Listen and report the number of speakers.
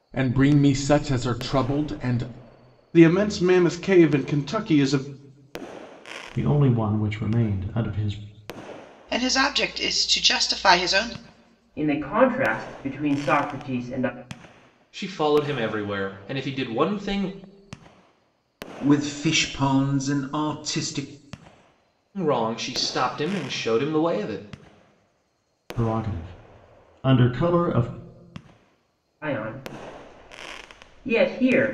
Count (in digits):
7